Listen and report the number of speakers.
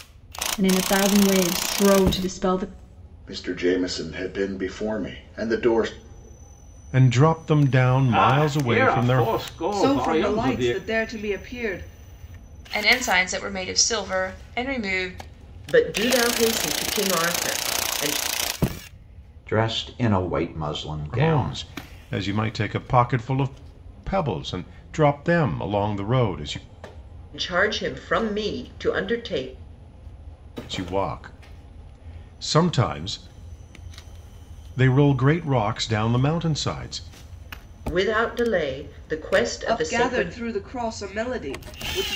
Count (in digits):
8